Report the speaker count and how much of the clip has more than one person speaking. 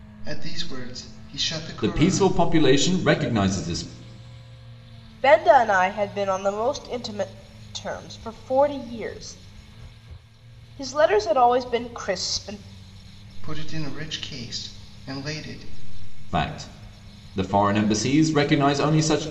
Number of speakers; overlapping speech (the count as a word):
three, about 3%